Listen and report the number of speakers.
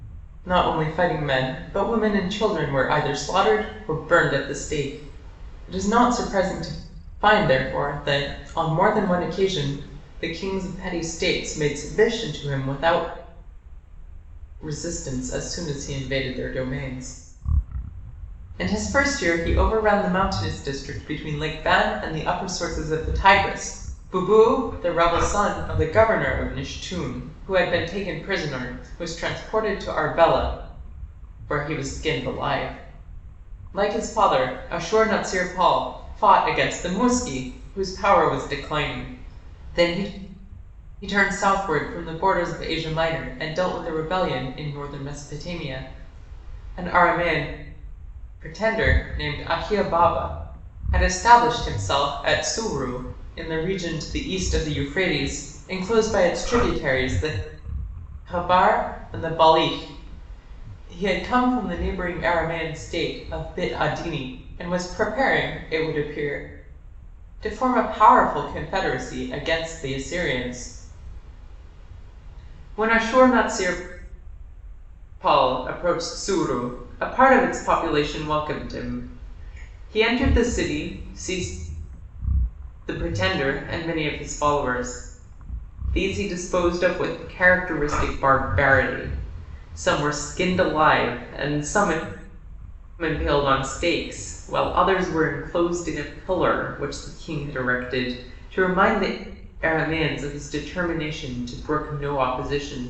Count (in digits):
1